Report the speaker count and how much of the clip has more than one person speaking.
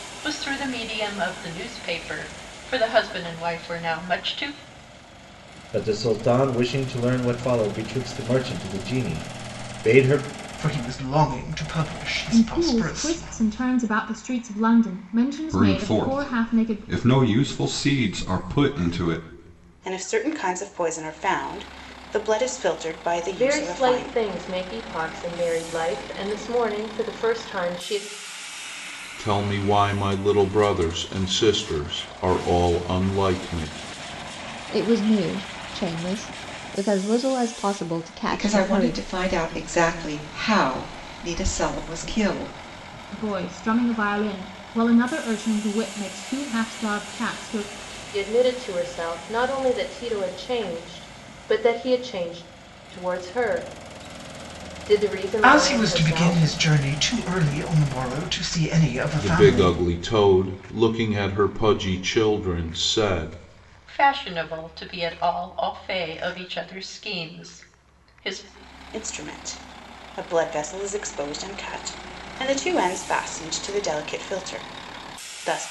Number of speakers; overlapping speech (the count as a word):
ten, about 8%